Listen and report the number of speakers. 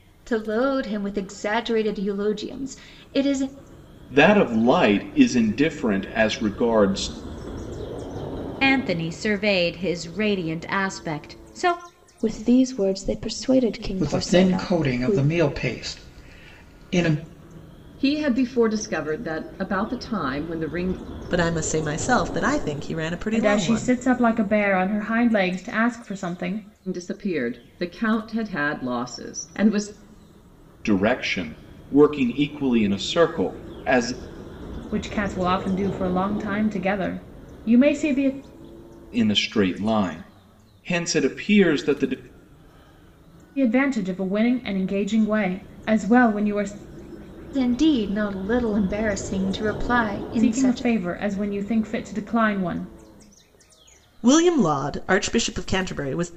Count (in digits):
8